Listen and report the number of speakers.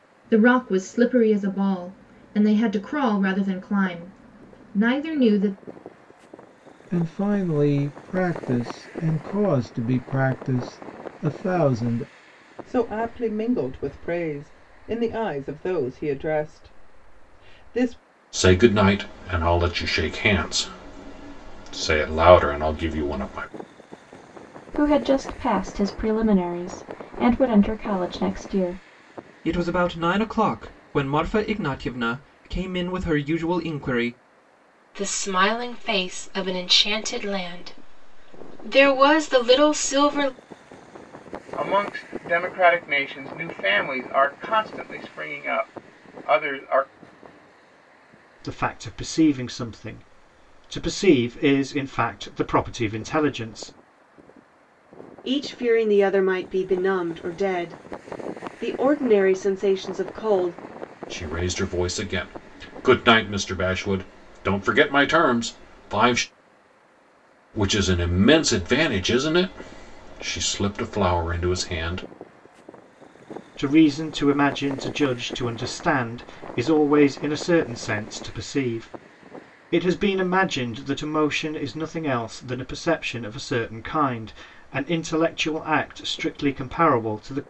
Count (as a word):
ten